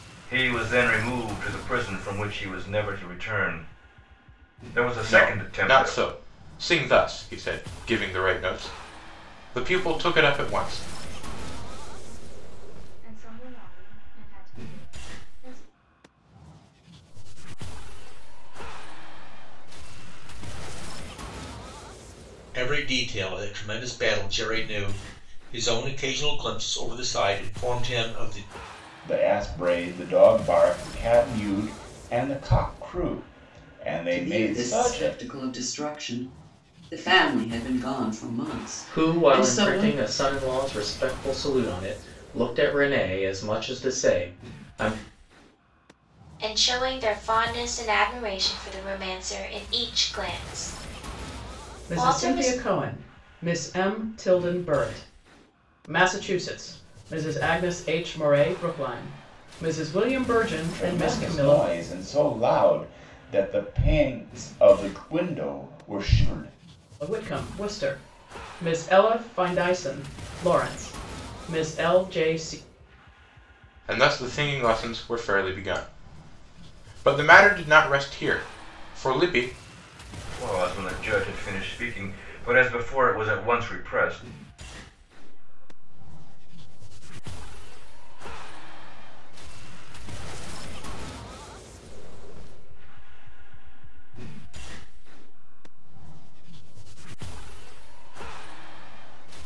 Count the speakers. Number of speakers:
ten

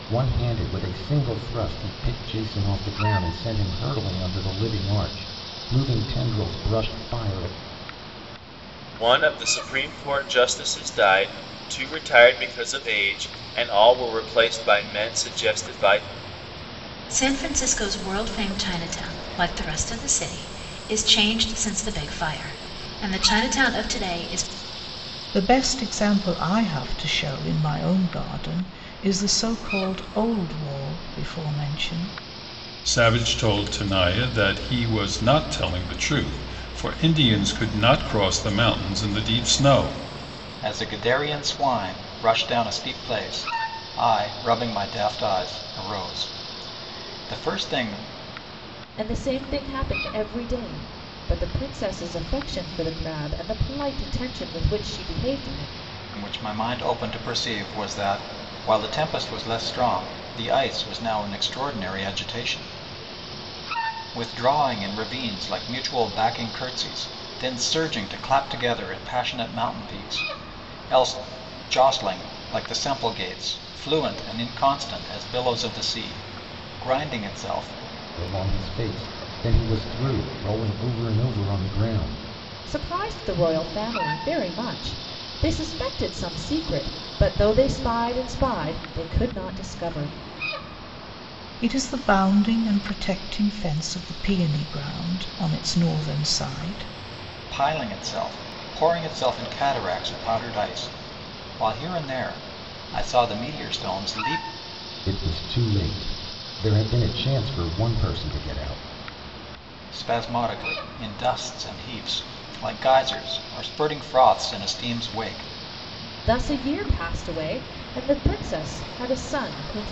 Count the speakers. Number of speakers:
seven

